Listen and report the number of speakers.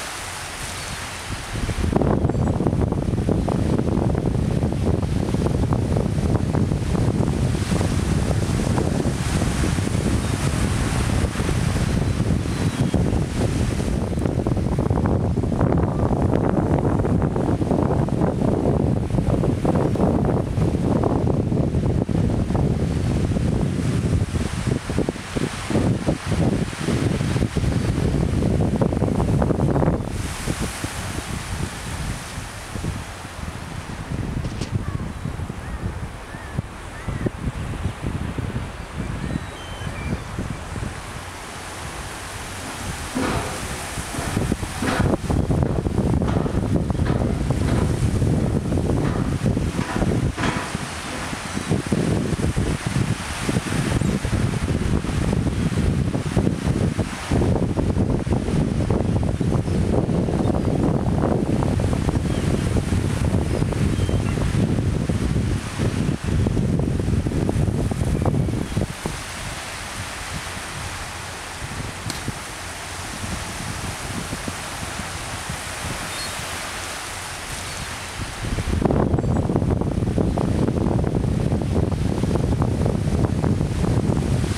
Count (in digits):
0